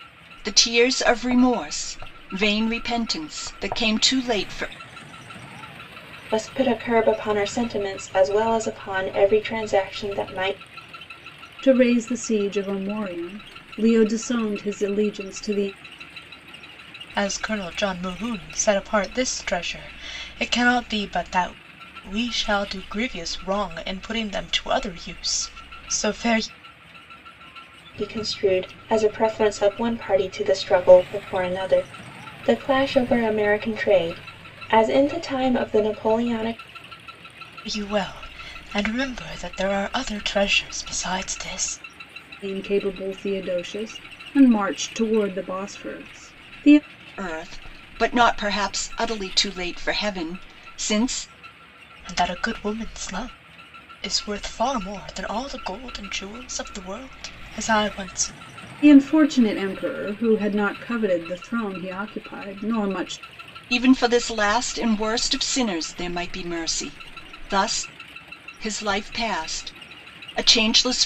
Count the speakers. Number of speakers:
4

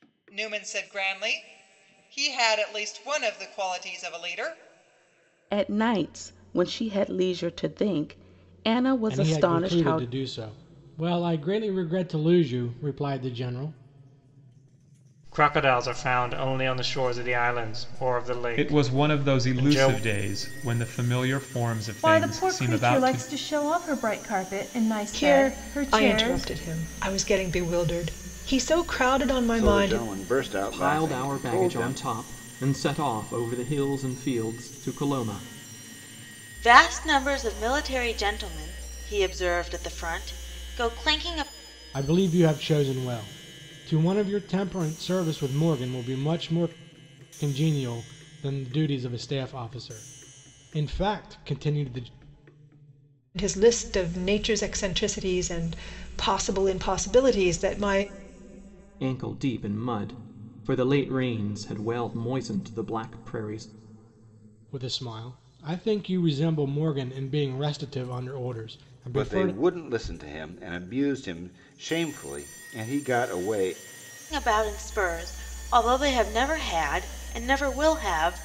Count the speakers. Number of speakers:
10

